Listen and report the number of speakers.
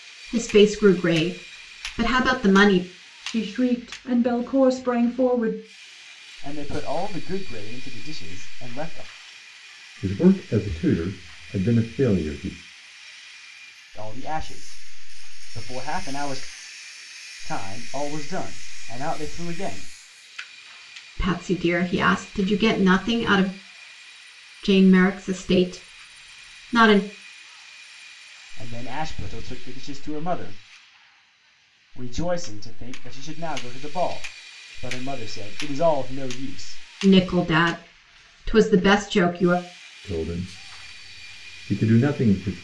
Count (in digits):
4